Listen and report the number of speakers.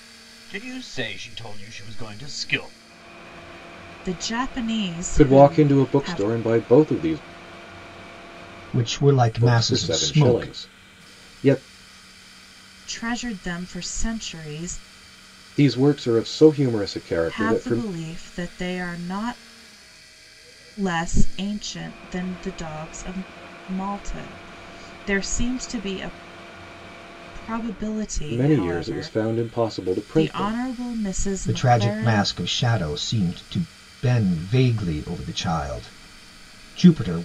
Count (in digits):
4